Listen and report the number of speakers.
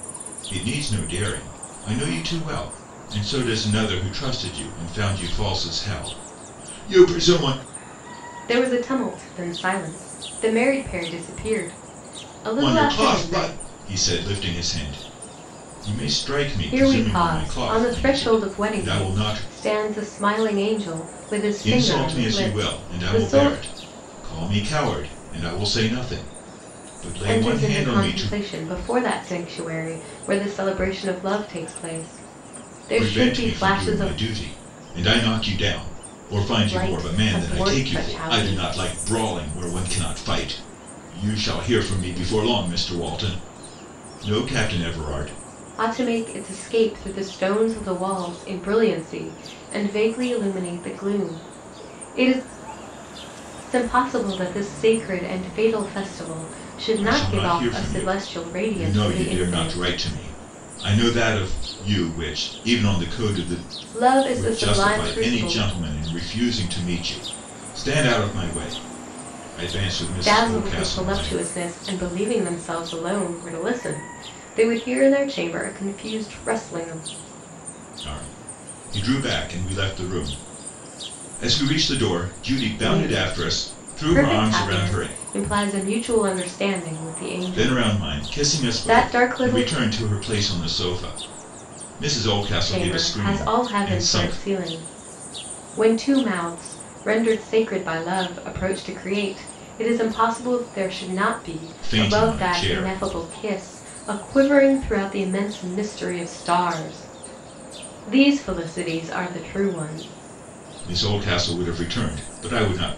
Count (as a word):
two